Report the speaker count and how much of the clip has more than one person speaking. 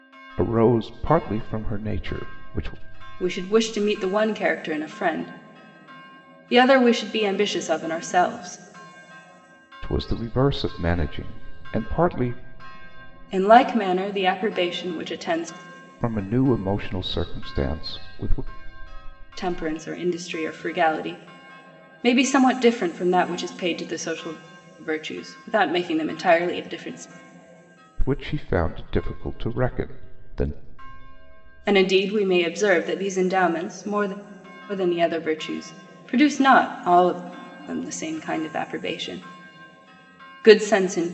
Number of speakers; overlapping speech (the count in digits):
2, no overlap